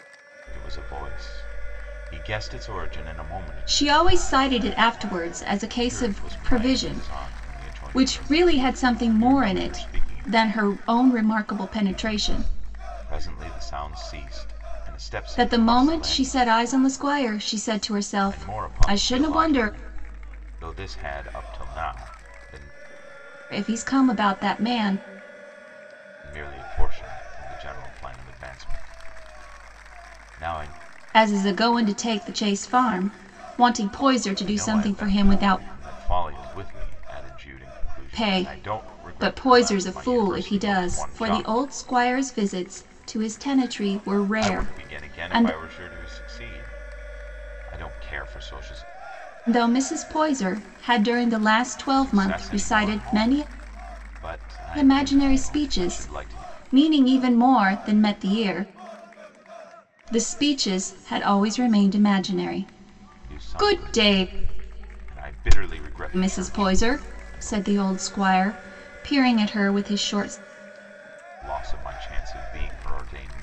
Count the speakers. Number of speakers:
two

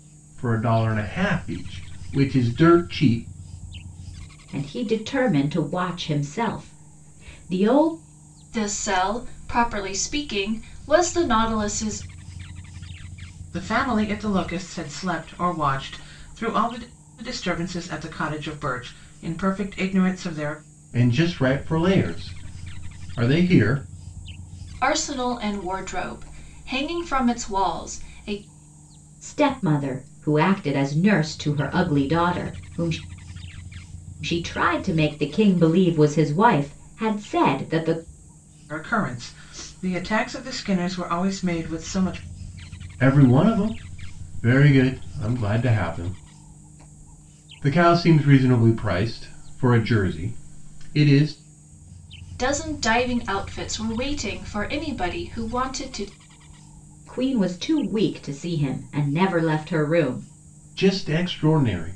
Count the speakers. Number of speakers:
four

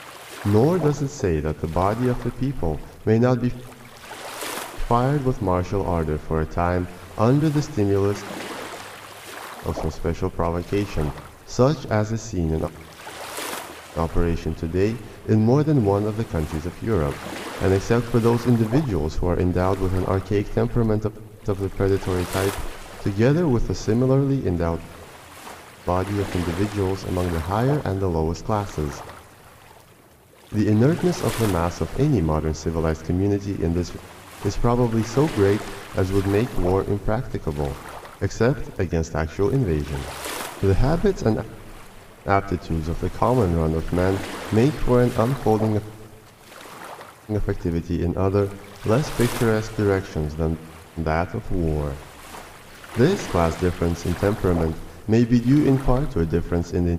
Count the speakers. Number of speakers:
one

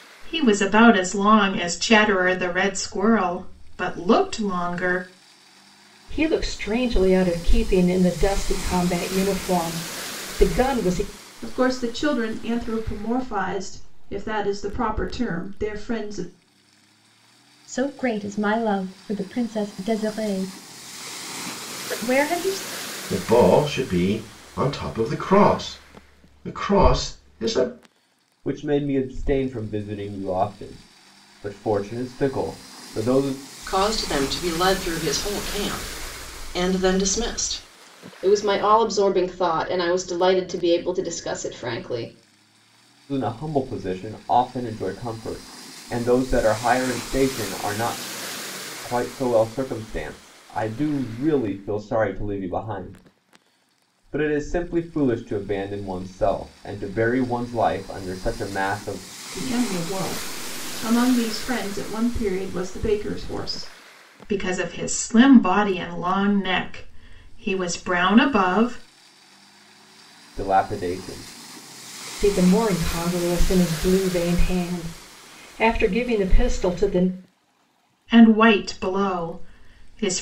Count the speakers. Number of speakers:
eight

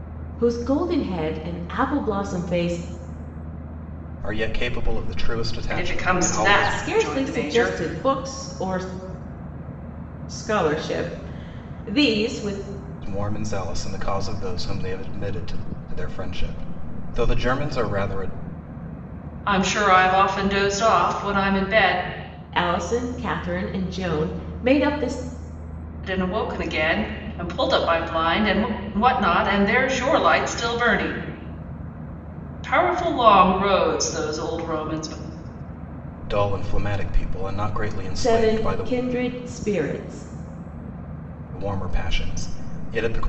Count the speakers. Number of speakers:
three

